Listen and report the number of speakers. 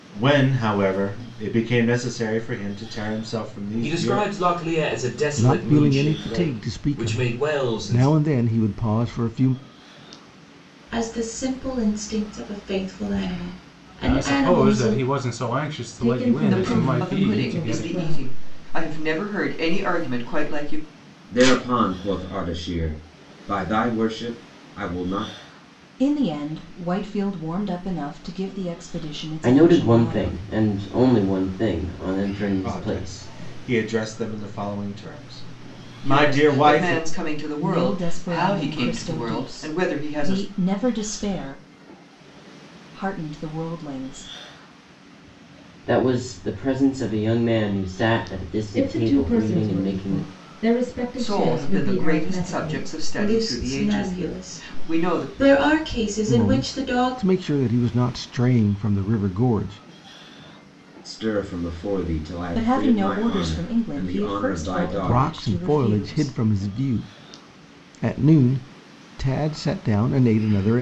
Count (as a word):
ten